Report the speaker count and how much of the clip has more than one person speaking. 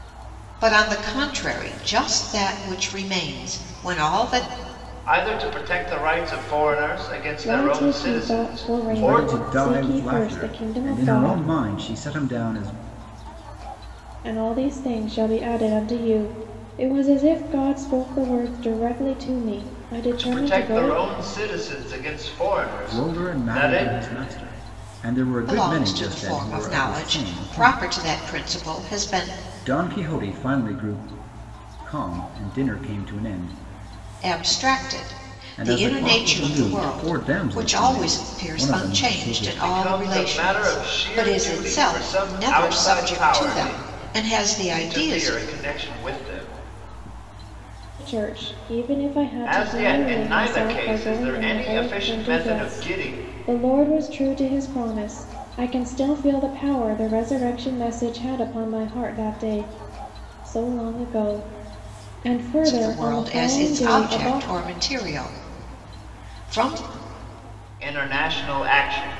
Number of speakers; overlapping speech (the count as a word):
four, about 35%